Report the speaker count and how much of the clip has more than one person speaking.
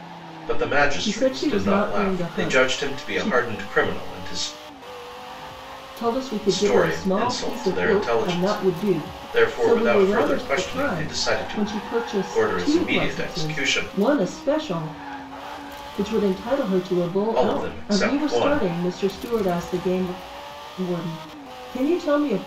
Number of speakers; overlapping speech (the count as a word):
two, about 44%